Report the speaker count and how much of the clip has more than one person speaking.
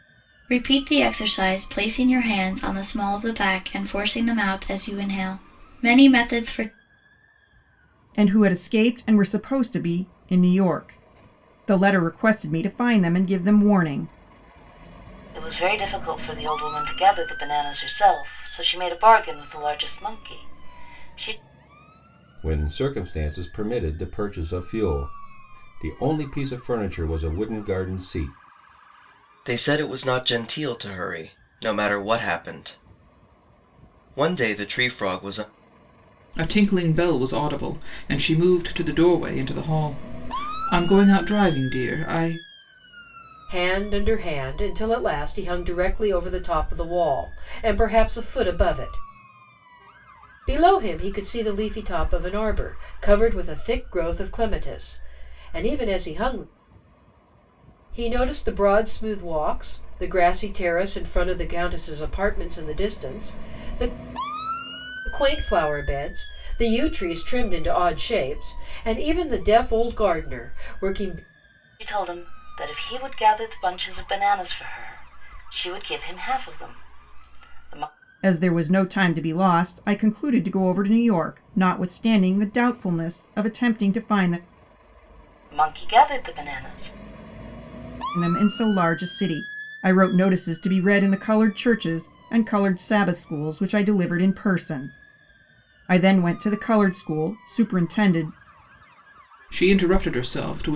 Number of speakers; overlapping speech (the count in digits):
7, no overlap